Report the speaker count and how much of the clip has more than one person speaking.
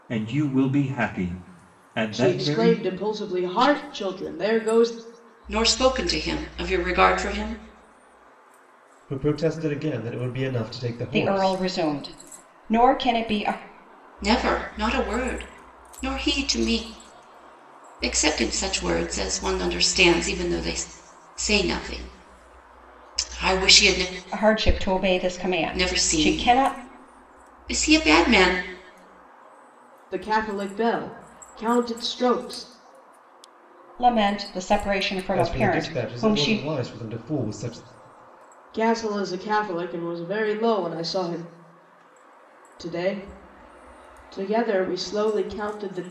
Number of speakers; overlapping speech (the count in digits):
5, about 8%